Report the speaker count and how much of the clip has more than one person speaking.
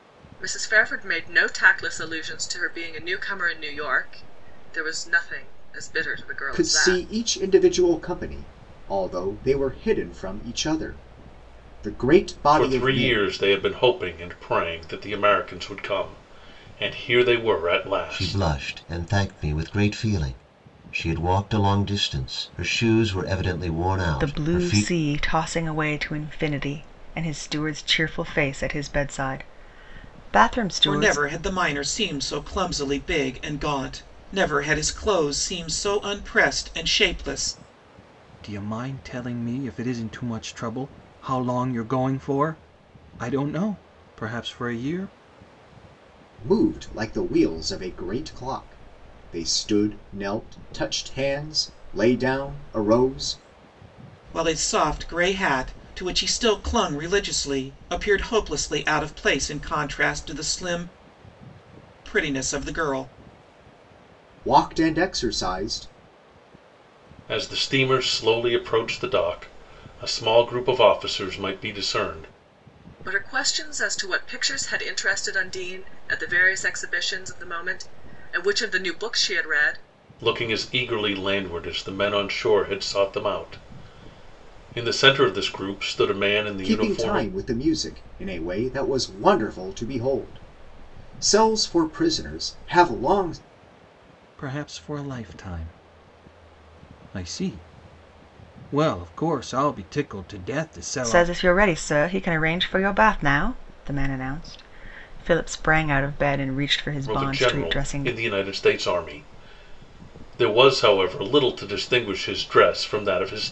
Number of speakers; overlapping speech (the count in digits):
7, about 5%